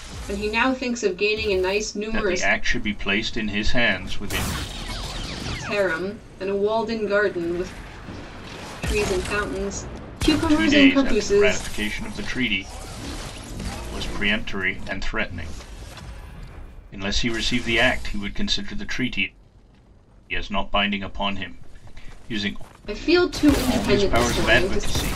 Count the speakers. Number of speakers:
2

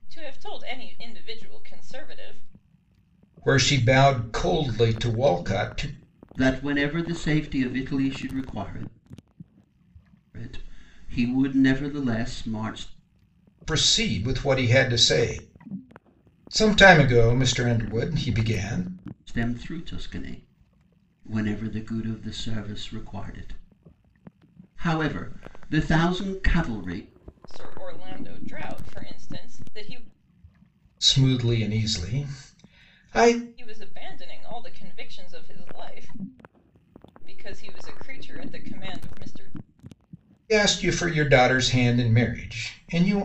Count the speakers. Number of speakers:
3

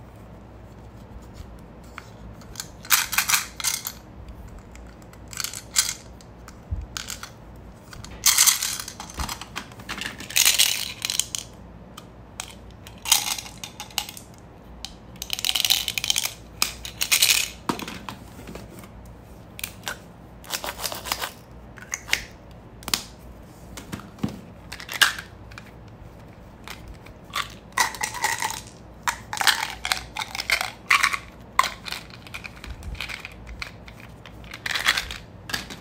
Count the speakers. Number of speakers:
0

